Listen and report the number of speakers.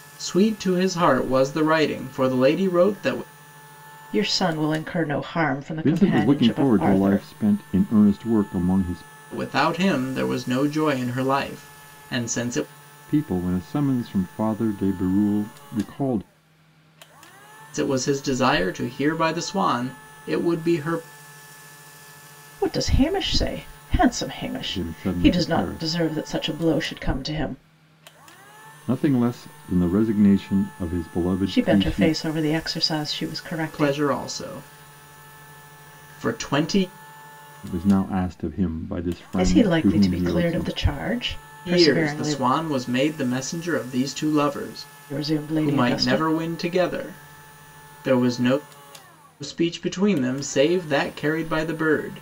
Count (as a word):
three